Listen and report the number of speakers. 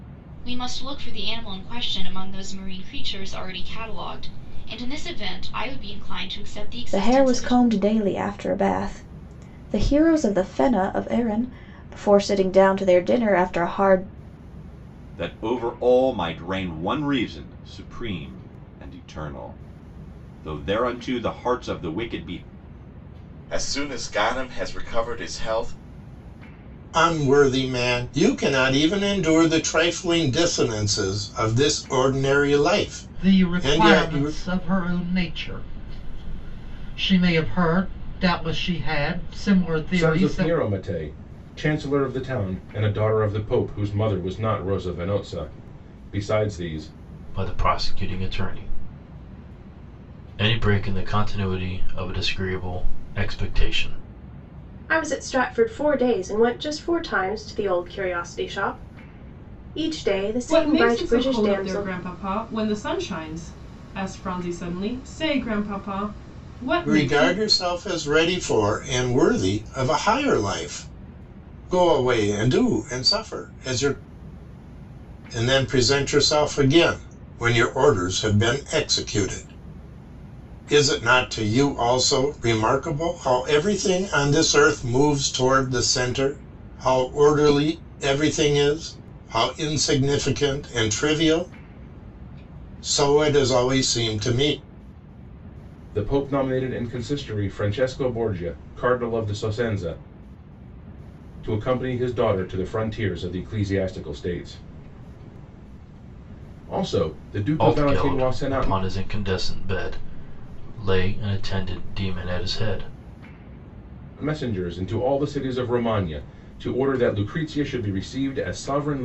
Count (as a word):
ten